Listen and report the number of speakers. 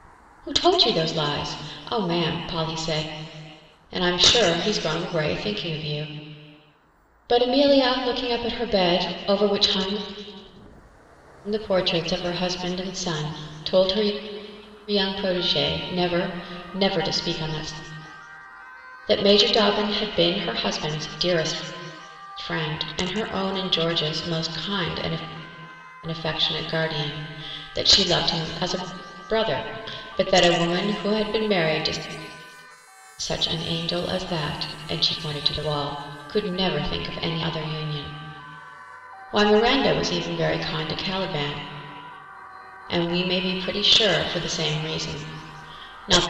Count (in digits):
1